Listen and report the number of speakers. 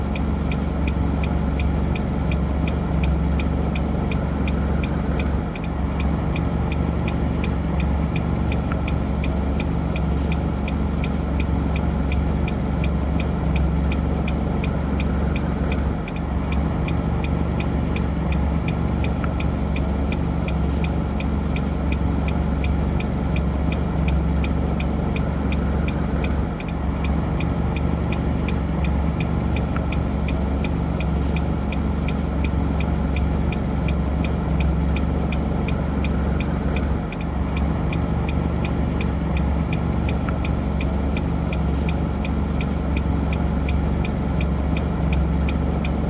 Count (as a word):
zero